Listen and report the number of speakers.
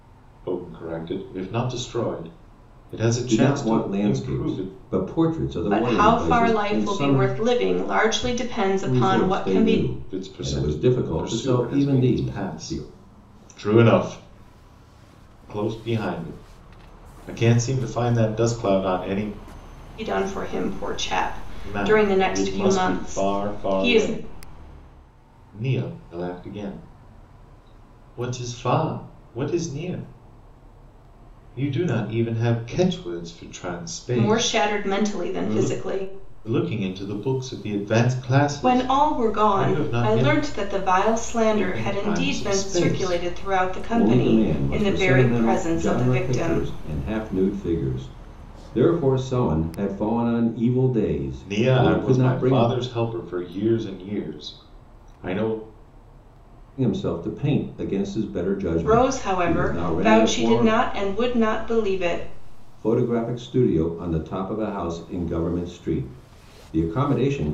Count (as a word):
three